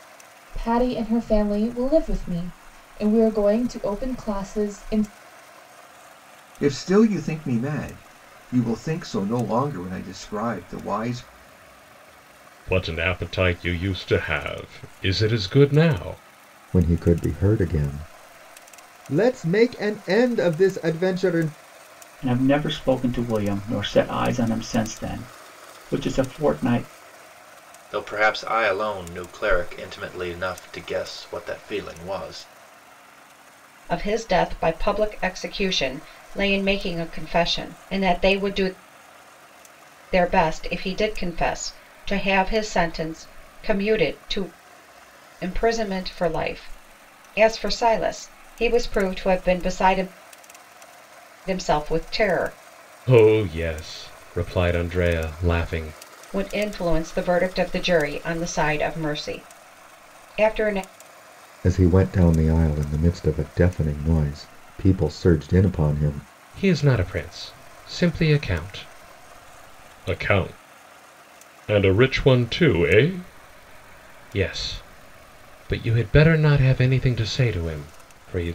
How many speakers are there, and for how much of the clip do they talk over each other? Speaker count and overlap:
7, no overlap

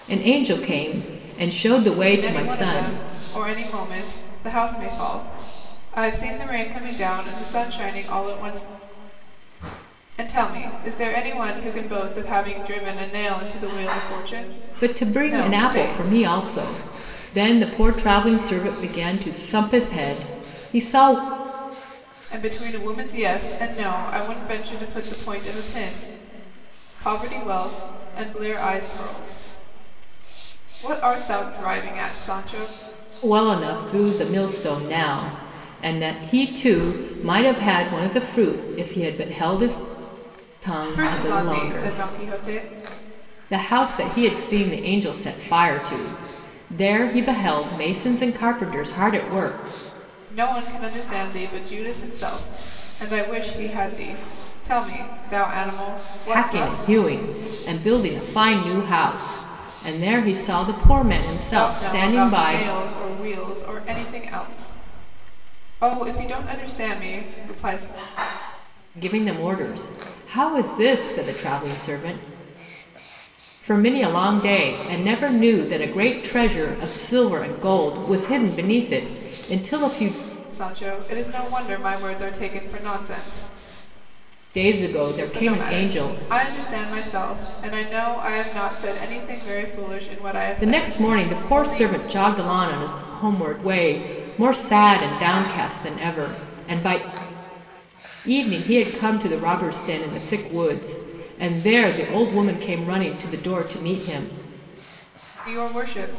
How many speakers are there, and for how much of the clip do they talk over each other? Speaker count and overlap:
2, about 7%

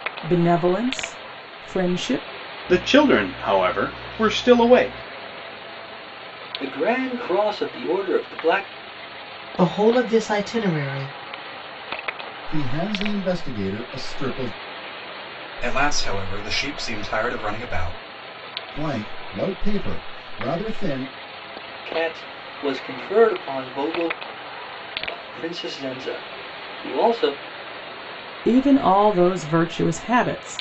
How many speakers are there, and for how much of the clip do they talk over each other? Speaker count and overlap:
6, no overlap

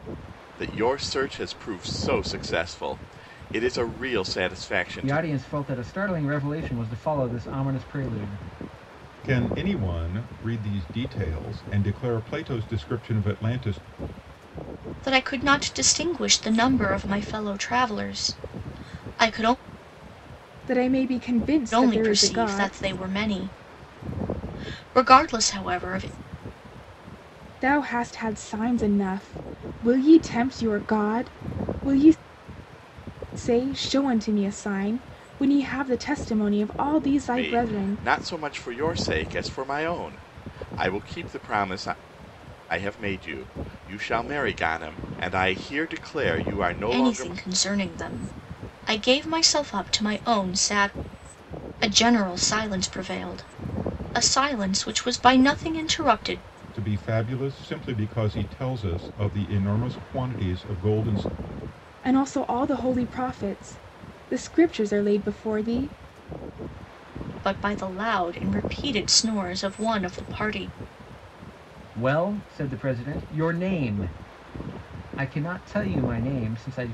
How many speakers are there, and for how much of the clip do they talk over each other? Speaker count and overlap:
5, about 3%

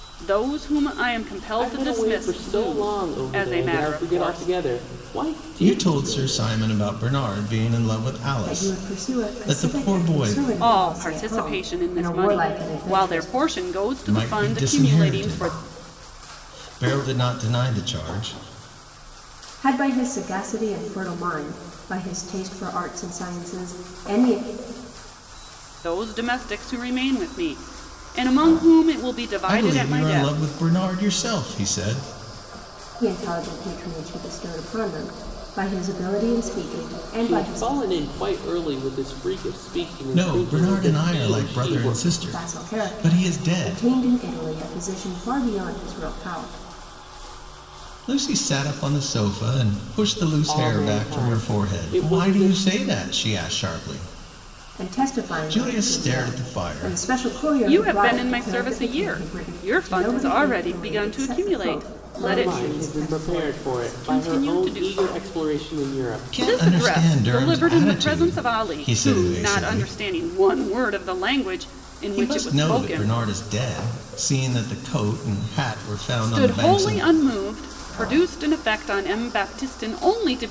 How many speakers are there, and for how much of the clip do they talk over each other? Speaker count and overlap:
4, about 42%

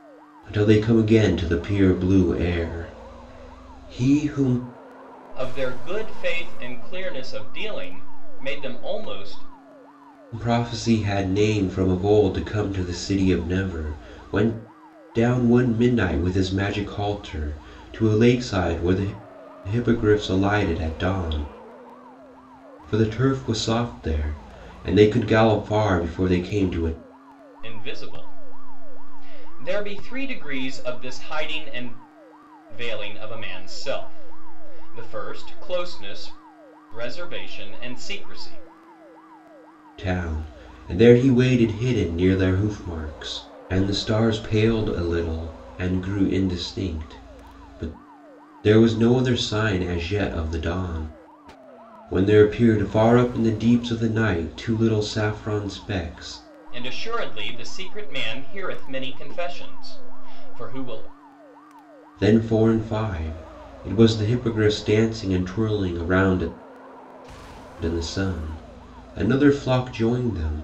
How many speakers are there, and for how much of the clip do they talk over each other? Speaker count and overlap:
2, no overlap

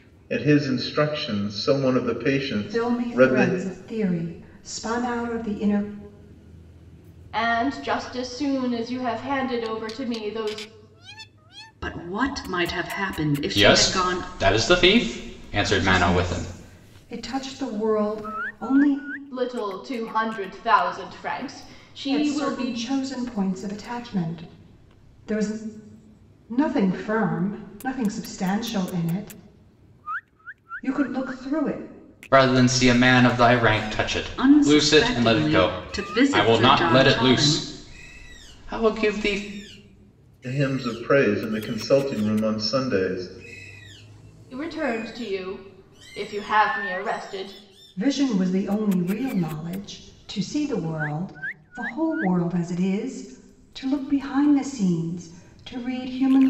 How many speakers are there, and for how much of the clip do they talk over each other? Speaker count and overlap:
5, about 11%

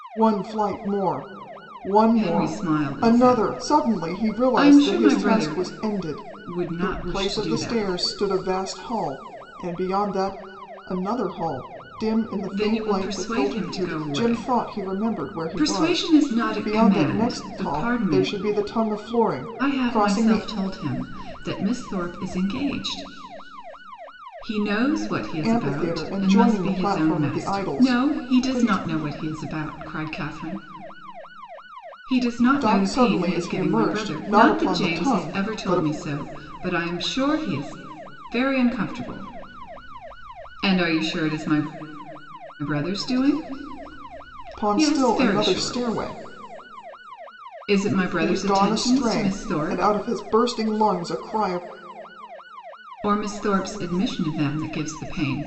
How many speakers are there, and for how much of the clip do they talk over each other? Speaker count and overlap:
2, about 37%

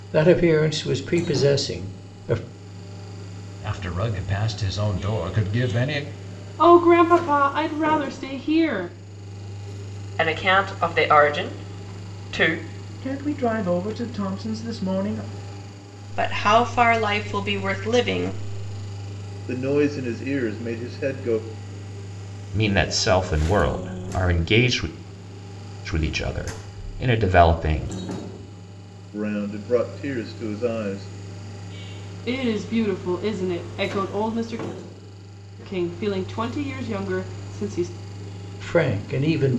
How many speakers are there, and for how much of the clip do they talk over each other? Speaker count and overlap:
8, no overlap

